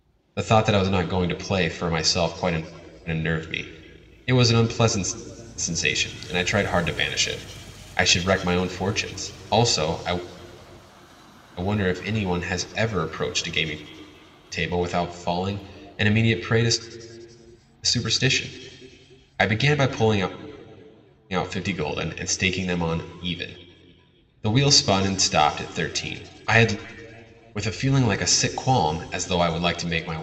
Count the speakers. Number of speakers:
1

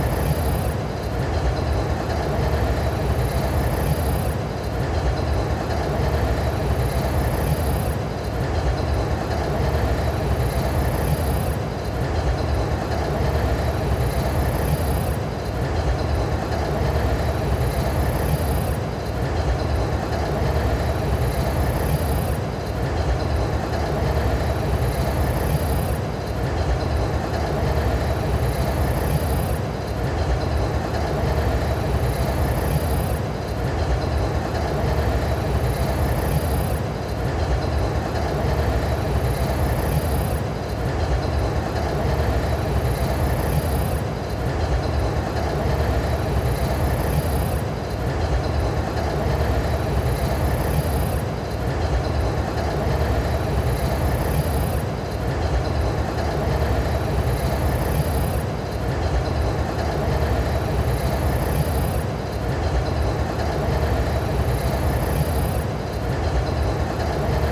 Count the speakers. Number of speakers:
0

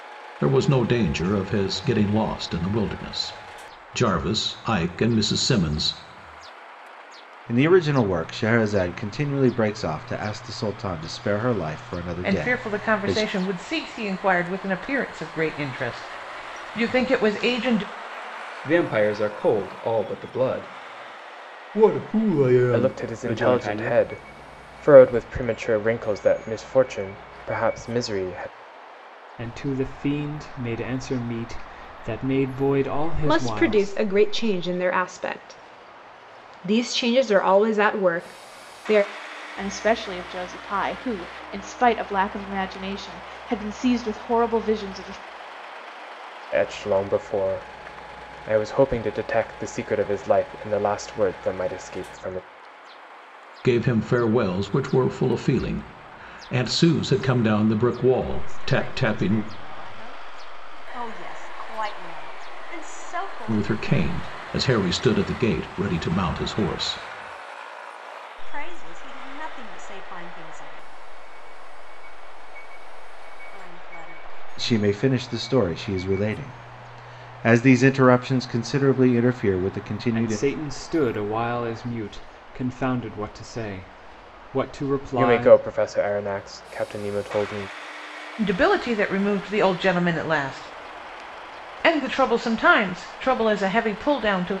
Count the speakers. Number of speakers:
9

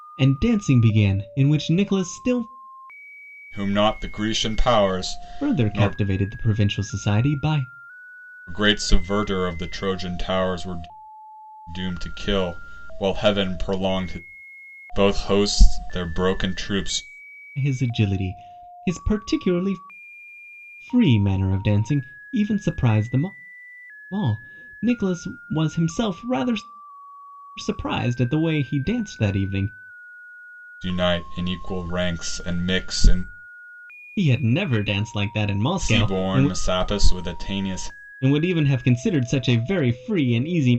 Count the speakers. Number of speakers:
2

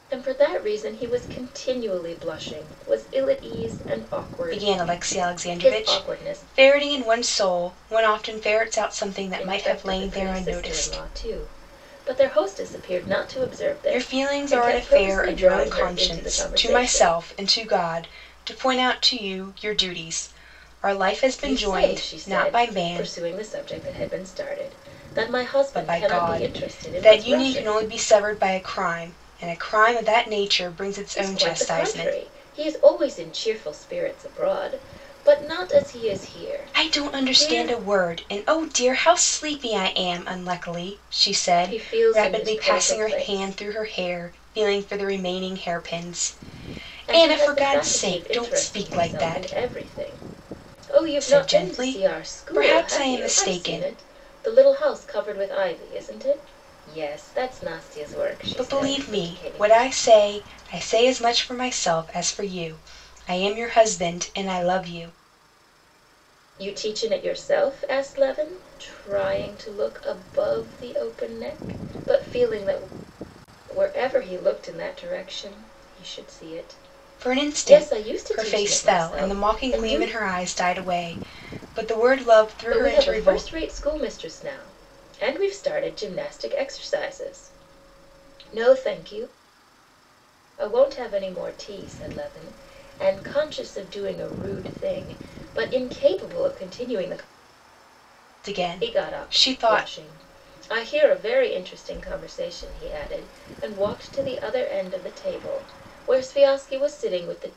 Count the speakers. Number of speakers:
2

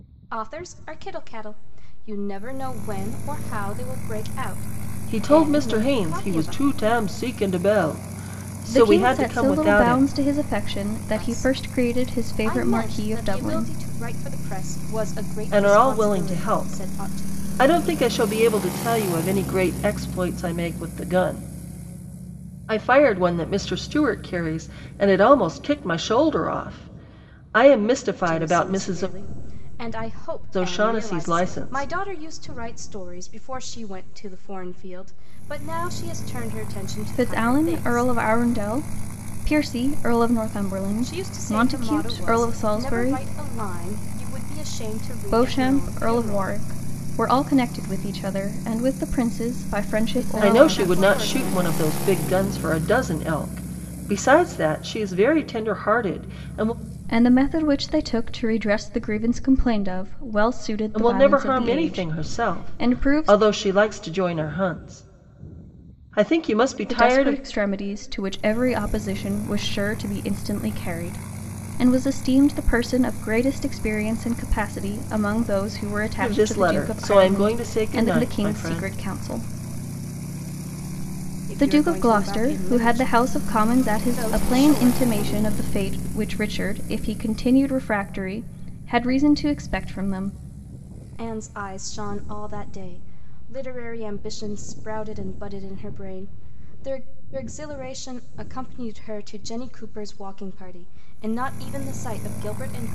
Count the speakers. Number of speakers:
3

